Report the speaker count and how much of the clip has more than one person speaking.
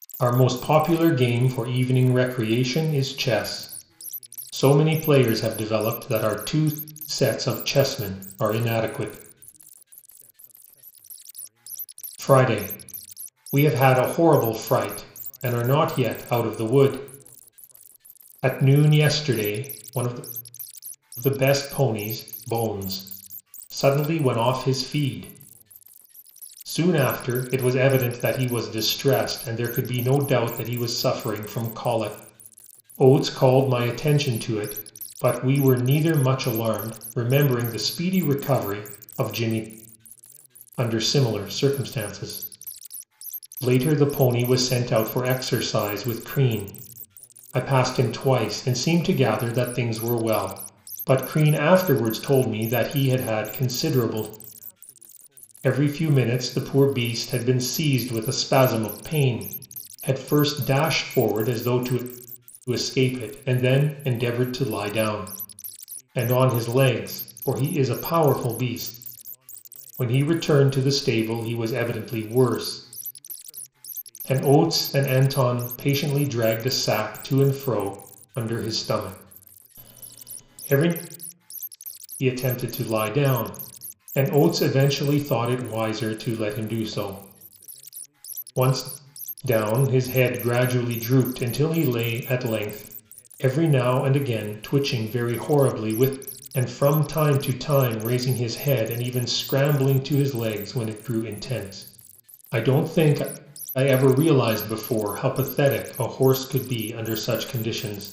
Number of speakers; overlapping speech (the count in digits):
1, no overlap